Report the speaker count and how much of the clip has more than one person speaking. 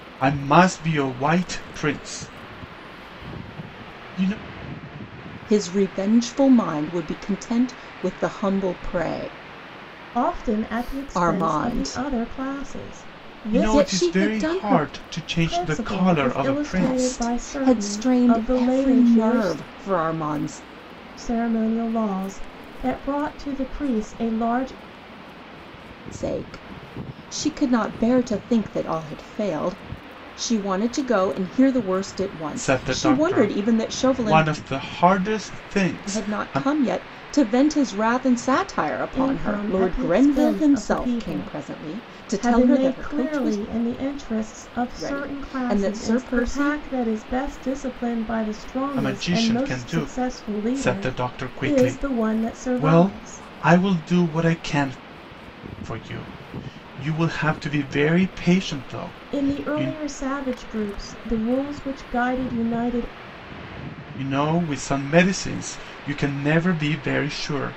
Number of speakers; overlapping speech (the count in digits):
3, about 30%